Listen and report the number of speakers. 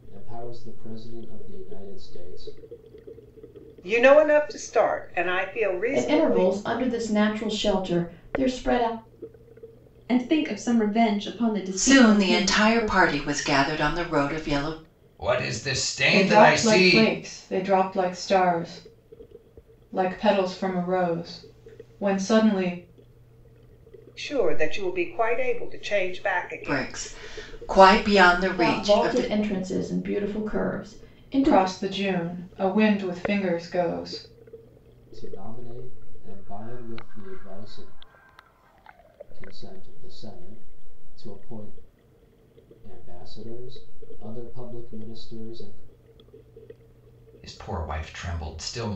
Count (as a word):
seven